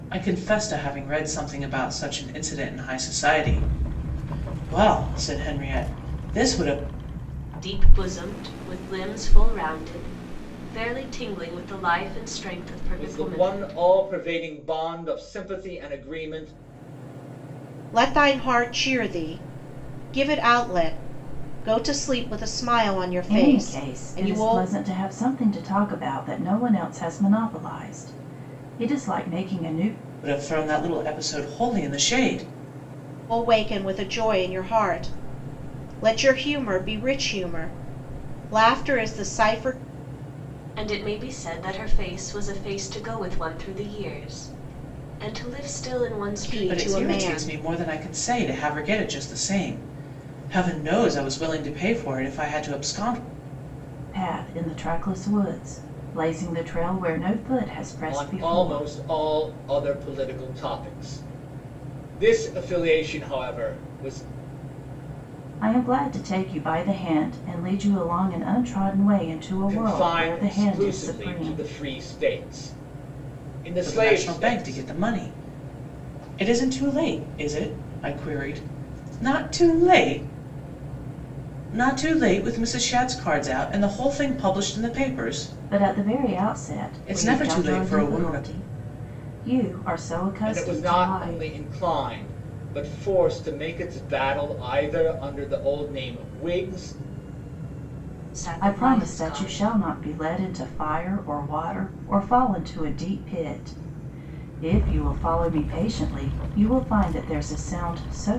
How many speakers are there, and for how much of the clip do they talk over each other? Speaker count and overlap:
5, about 11%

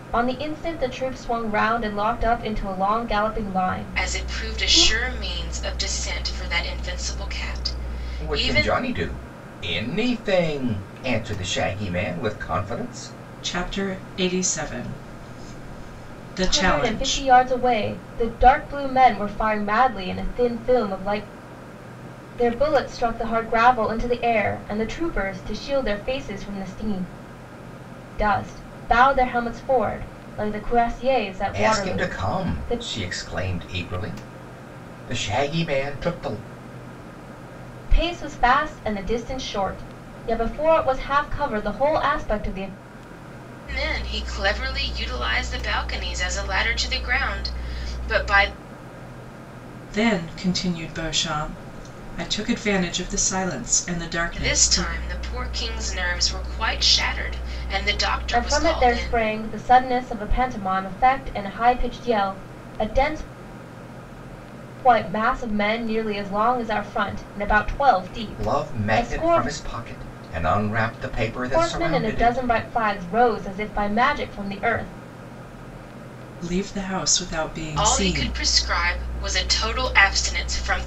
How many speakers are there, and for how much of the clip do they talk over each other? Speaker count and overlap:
4, about 10%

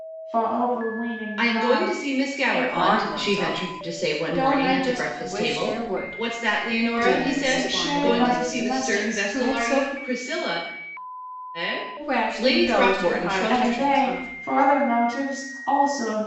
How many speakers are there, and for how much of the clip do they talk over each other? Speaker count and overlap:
3, about 64%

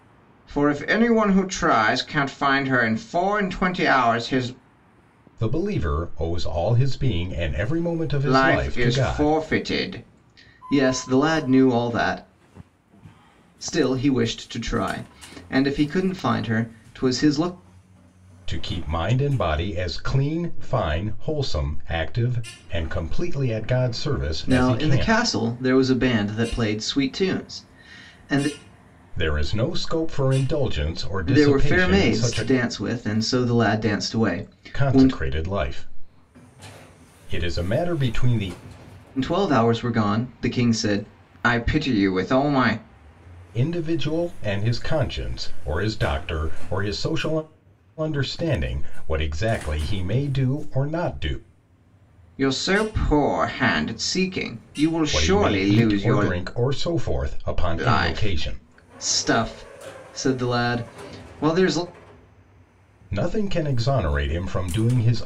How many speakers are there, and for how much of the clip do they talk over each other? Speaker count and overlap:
2, about 9%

